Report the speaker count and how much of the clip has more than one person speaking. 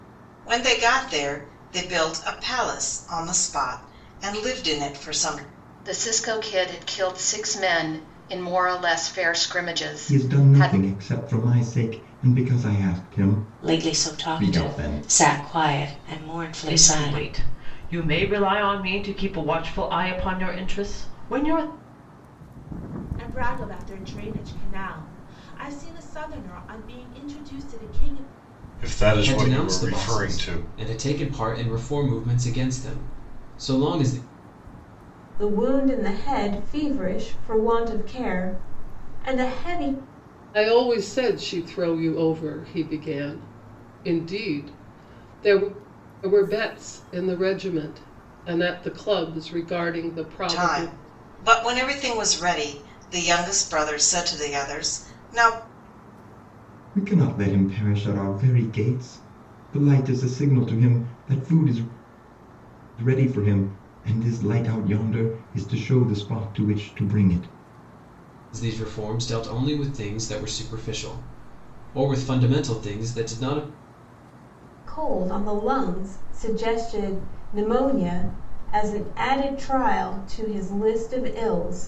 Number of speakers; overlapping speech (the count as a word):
ten, about 6%